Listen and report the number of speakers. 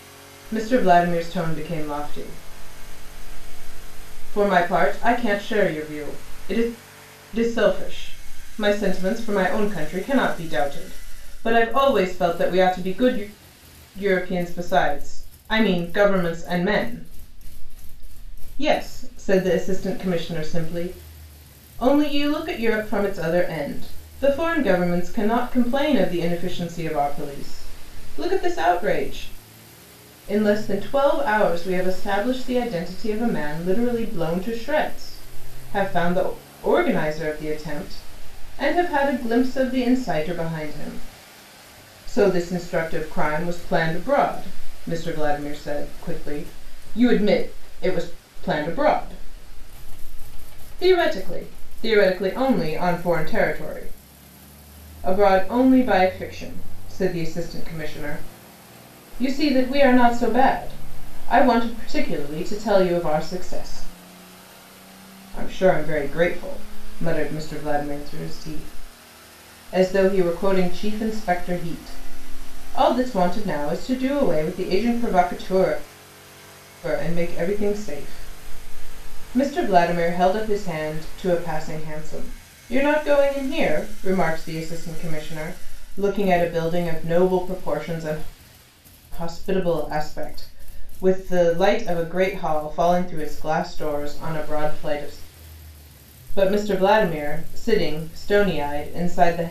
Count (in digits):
1